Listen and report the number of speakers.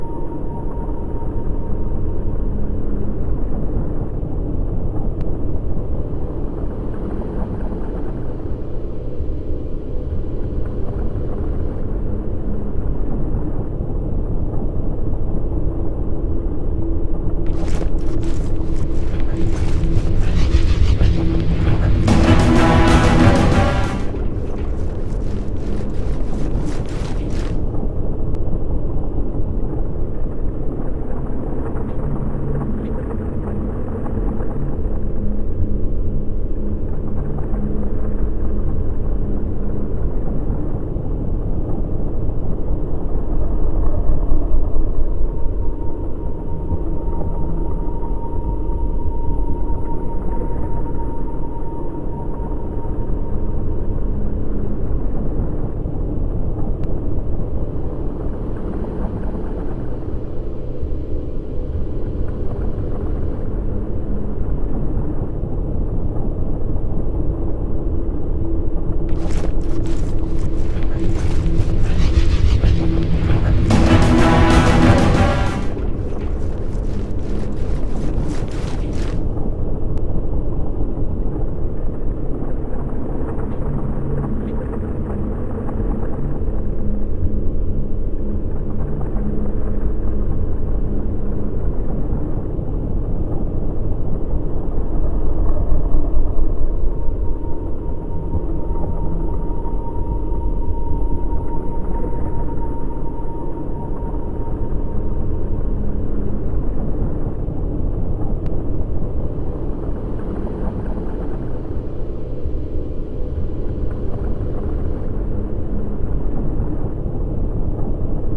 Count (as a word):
zero